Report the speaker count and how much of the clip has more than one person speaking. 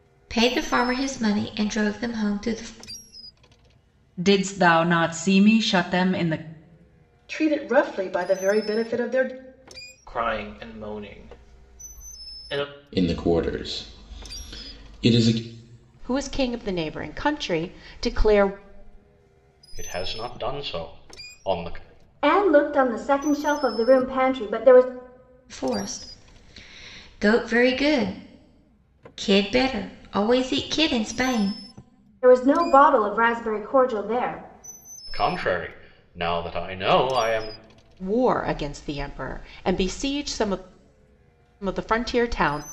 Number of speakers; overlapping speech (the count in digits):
8, no overlap